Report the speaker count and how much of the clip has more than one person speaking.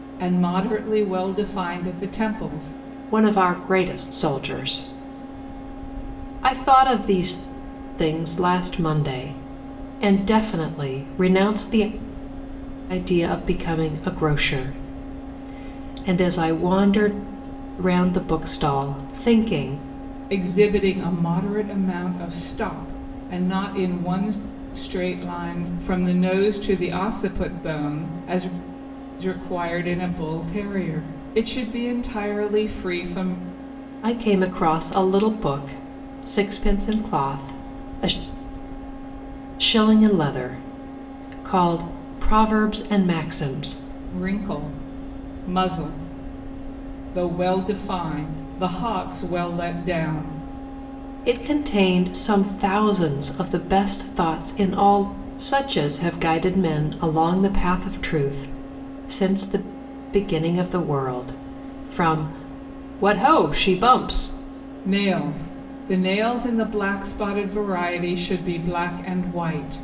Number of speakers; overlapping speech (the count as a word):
two, no overlap